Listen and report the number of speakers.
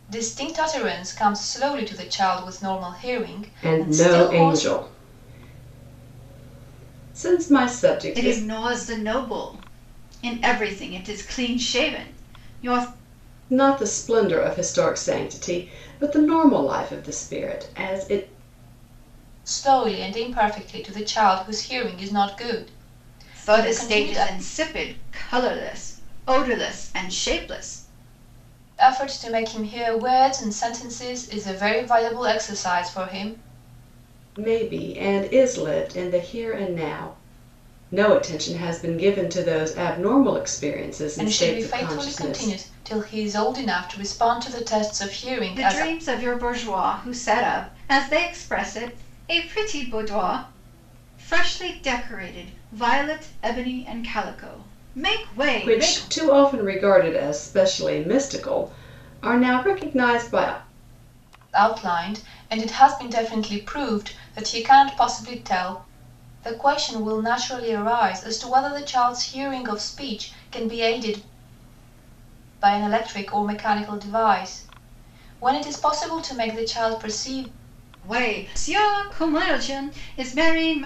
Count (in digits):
3